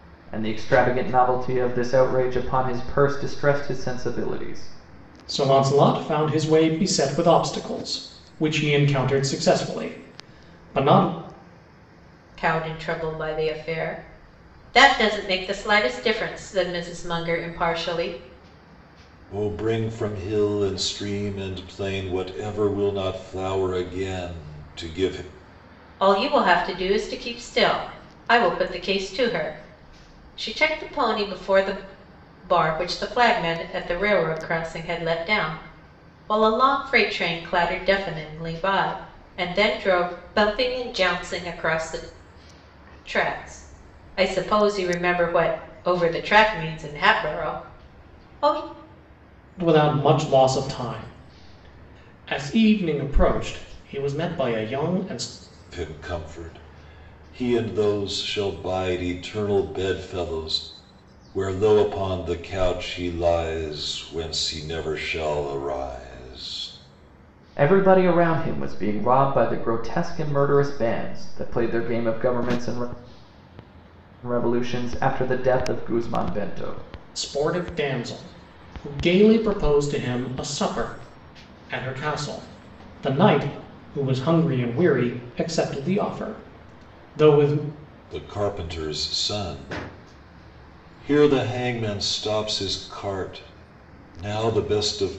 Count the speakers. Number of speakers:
4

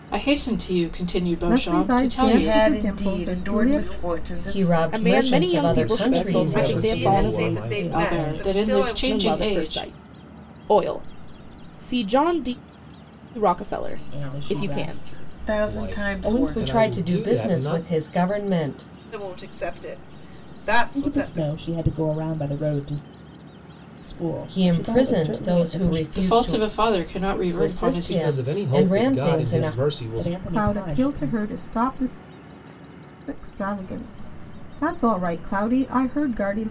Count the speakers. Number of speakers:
9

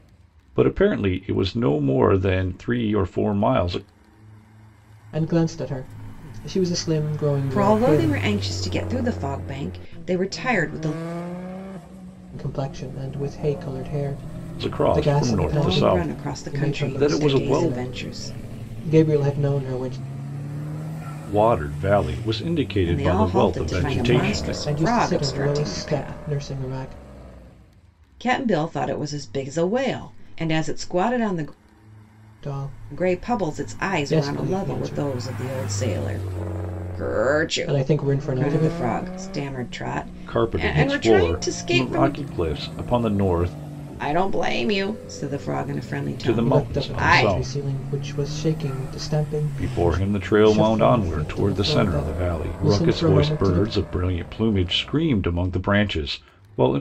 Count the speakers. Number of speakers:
3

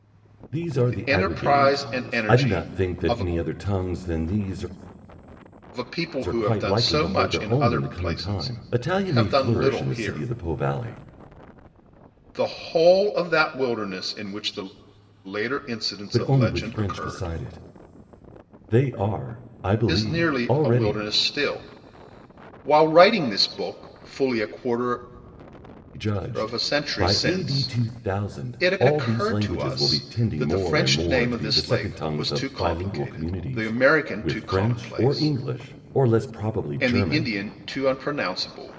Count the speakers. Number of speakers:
2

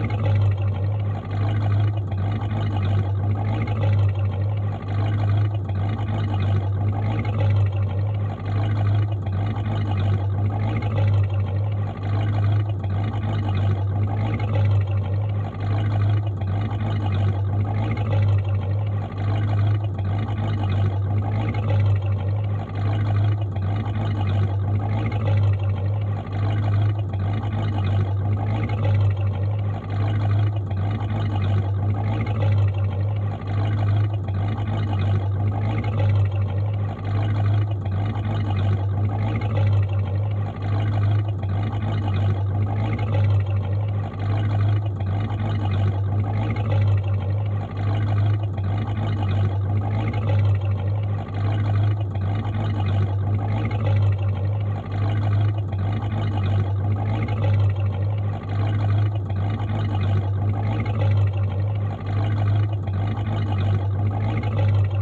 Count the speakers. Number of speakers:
0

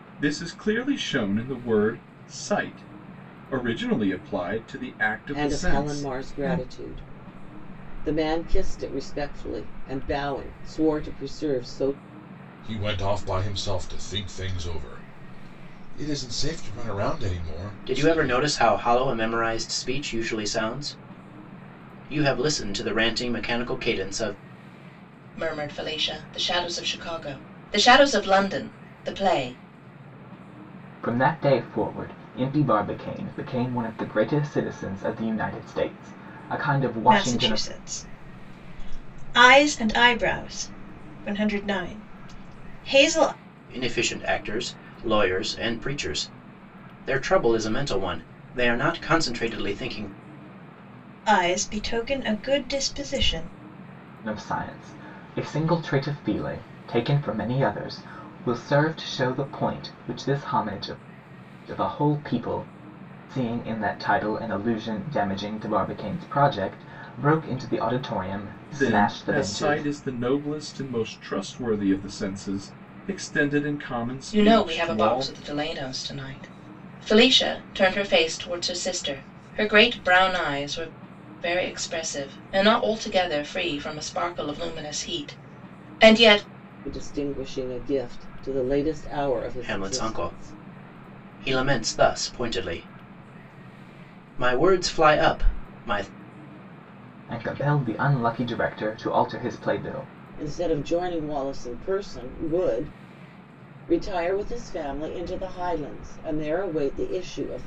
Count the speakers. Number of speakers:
7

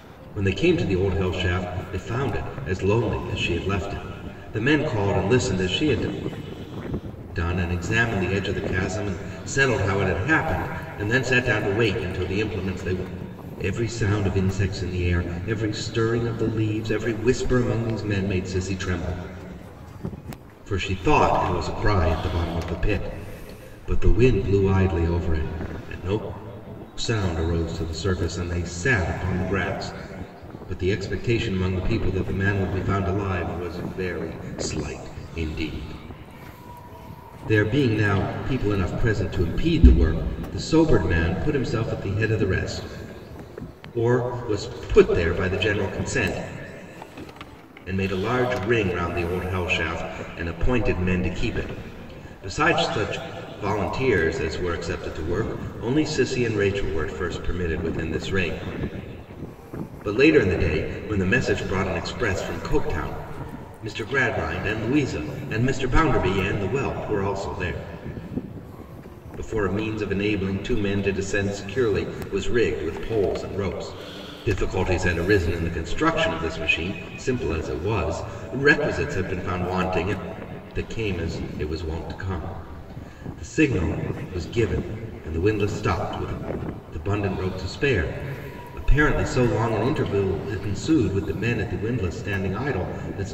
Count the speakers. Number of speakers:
1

